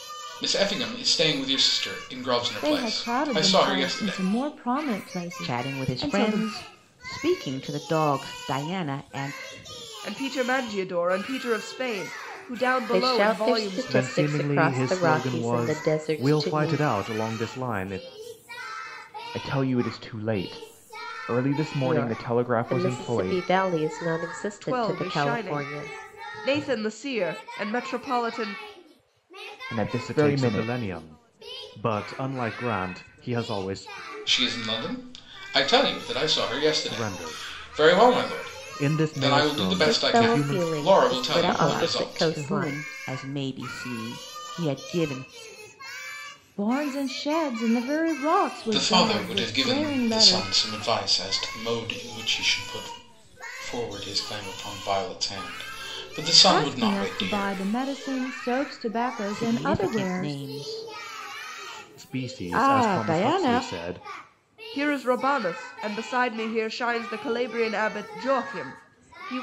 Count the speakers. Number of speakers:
7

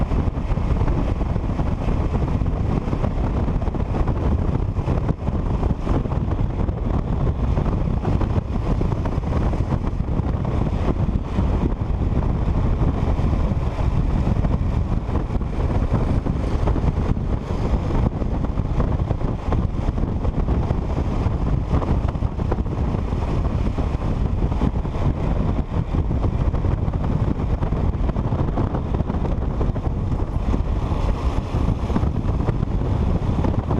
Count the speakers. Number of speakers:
0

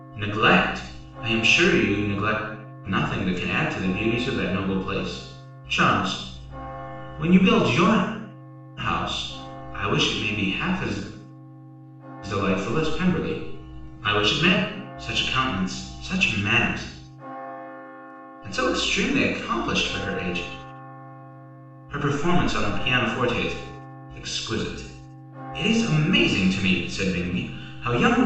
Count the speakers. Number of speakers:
1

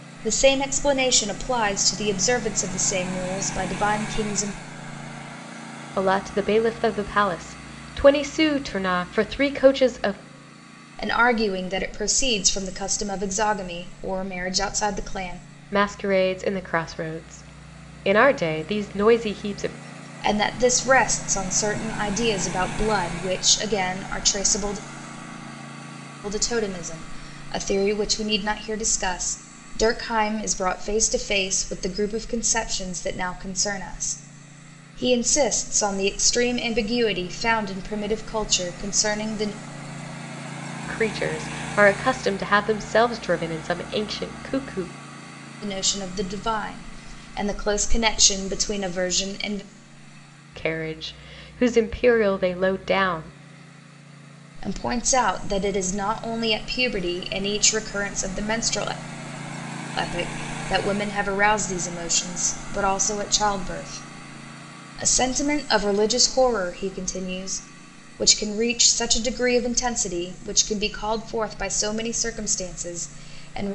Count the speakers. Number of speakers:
2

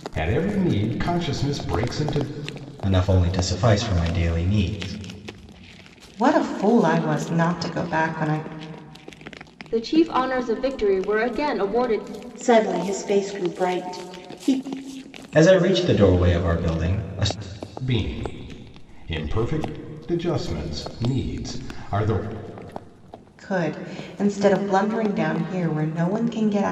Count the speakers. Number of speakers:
5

